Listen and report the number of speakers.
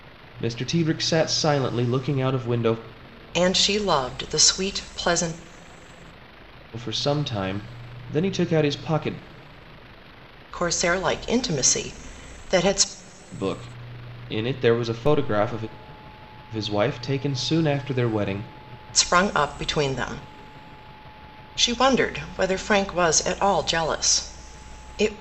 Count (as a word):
two